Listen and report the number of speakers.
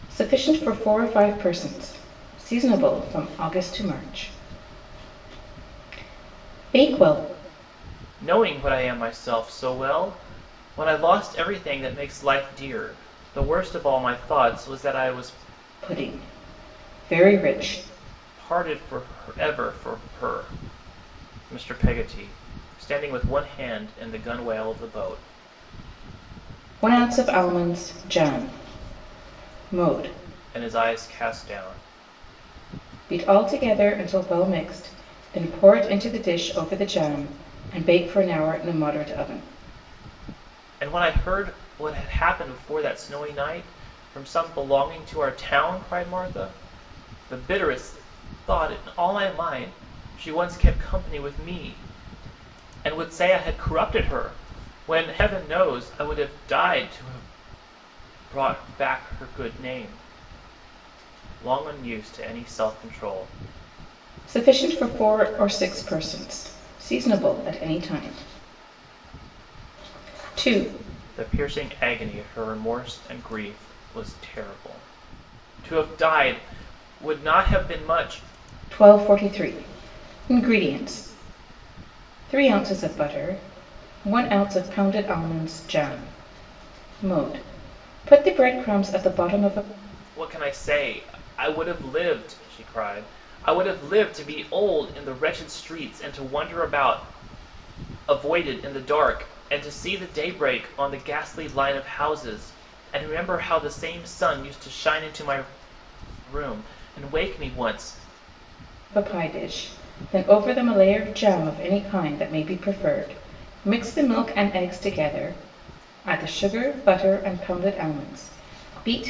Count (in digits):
2